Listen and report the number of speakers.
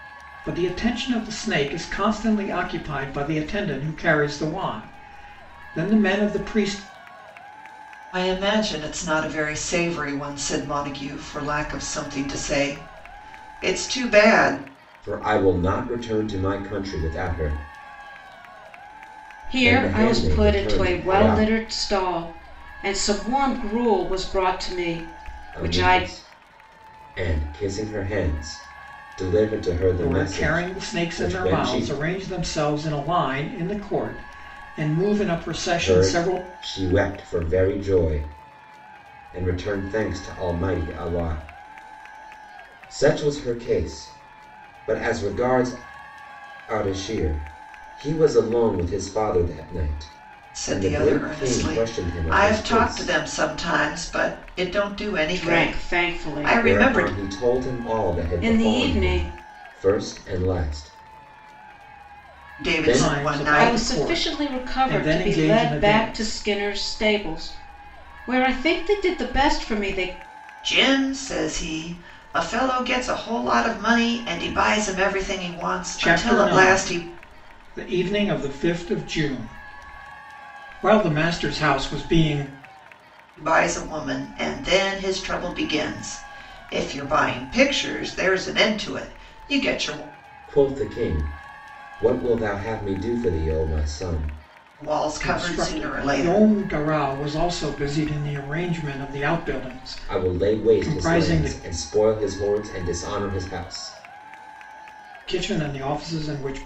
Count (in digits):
4